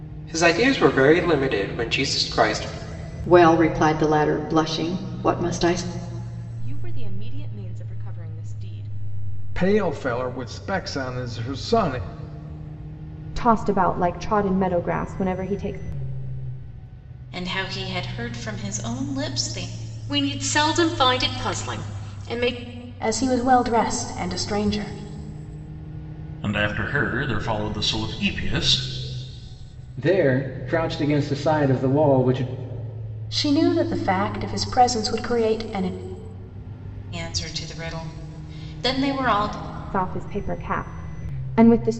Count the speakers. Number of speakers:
10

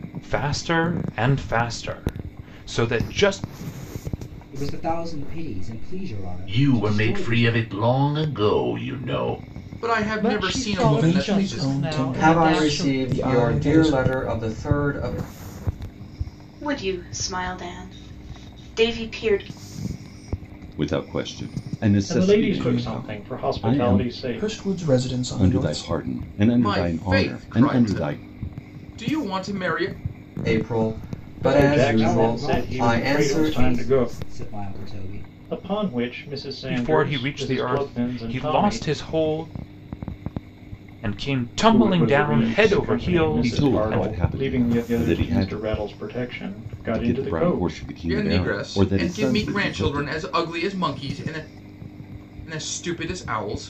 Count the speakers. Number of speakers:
10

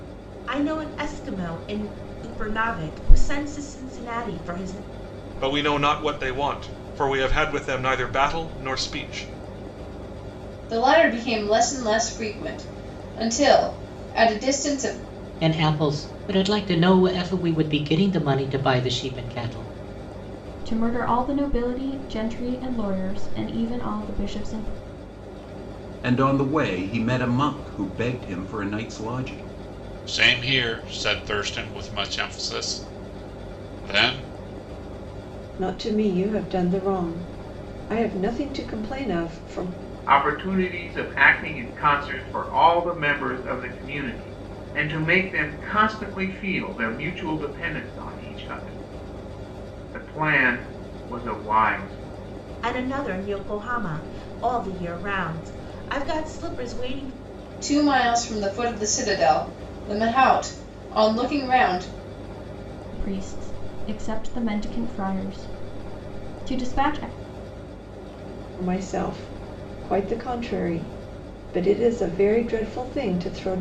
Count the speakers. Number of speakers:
9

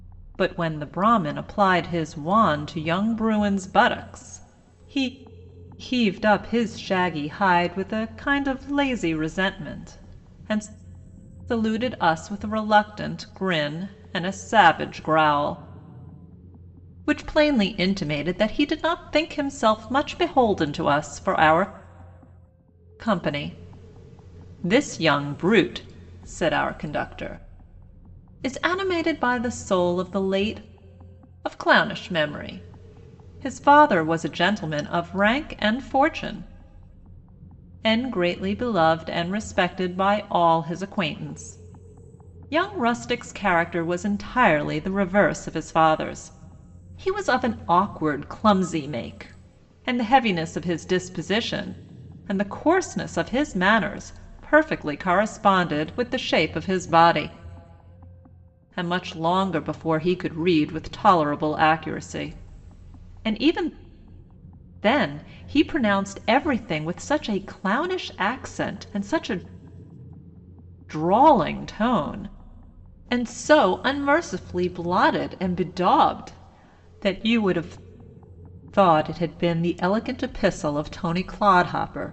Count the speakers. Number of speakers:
1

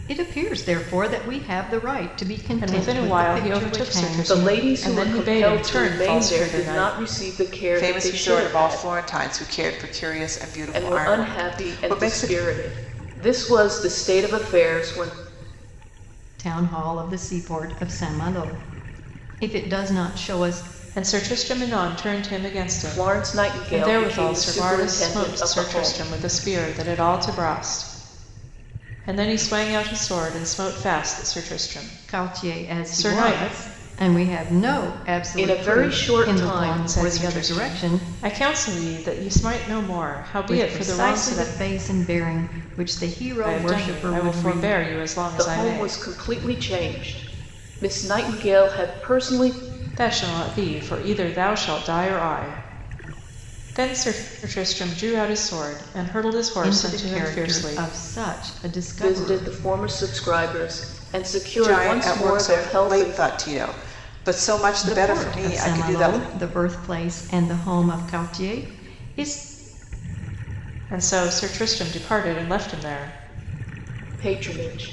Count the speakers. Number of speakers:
4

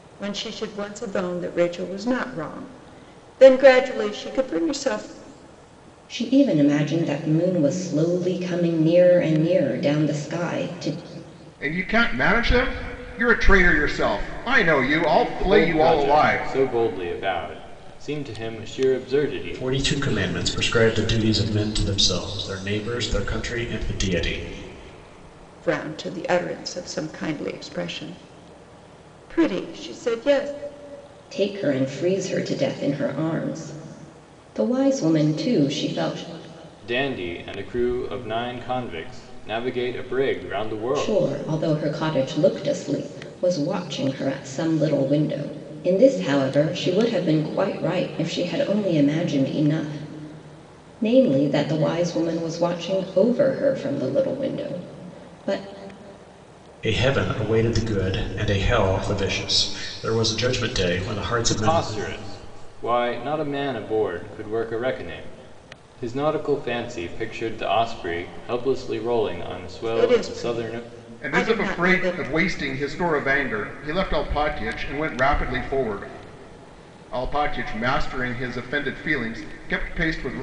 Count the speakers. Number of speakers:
5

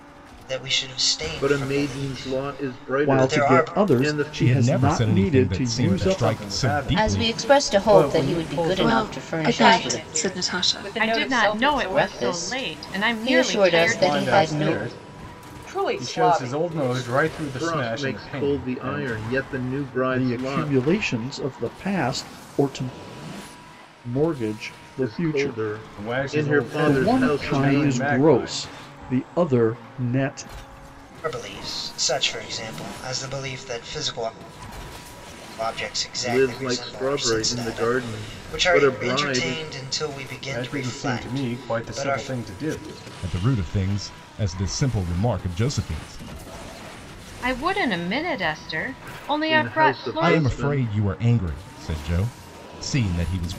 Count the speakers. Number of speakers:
9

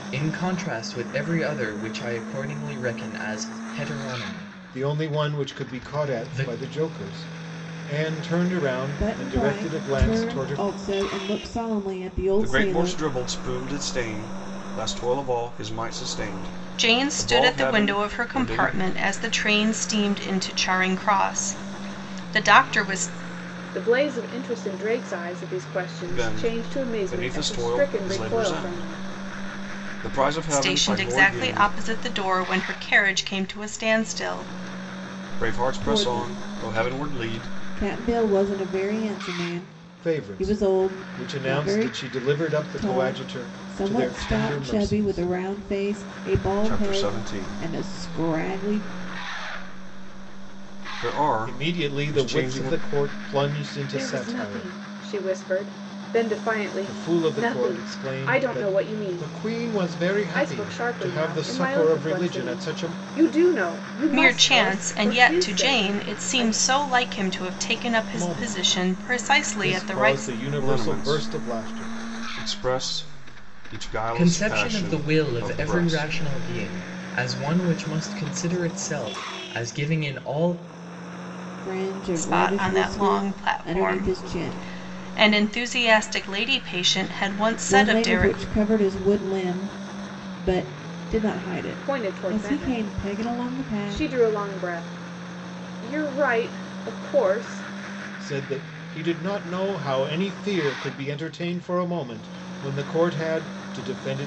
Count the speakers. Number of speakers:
6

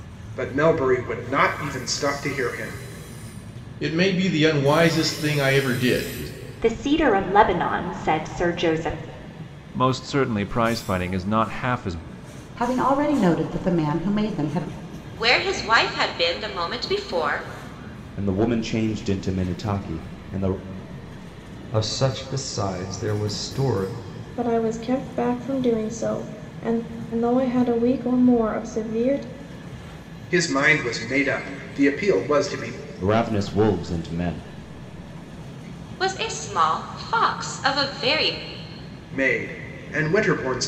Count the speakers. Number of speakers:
9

